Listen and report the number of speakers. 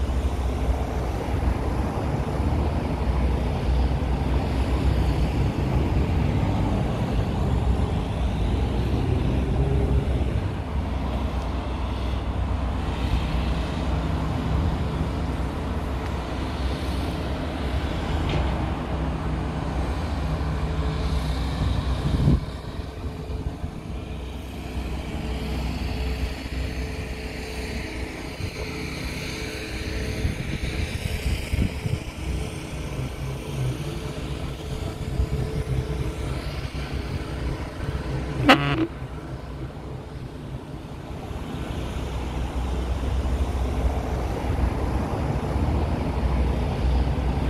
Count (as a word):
zero